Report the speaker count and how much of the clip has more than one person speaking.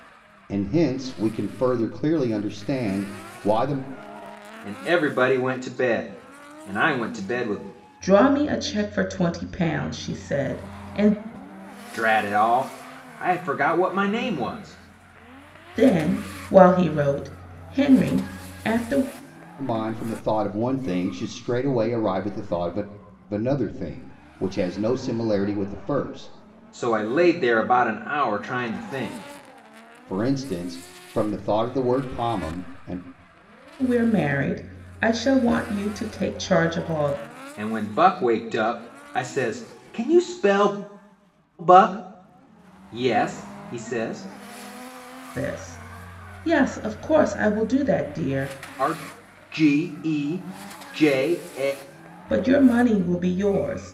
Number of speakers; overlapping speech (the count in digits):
3, no overlap